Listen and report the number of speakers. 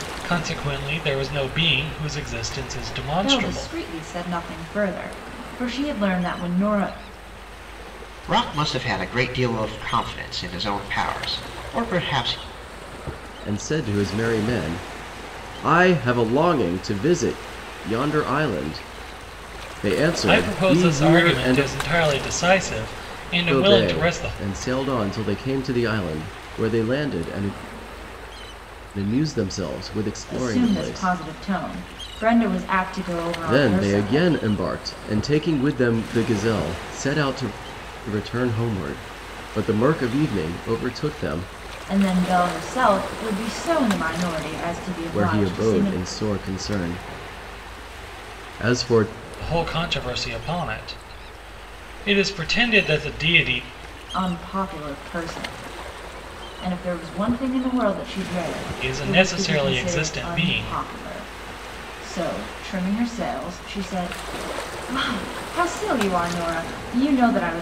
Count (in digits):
4